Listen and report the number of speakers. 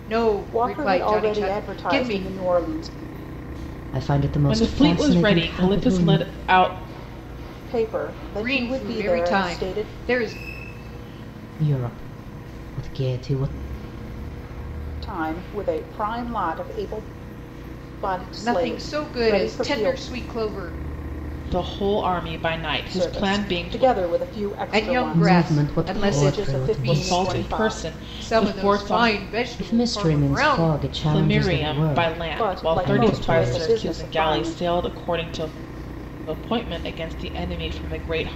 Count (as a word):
four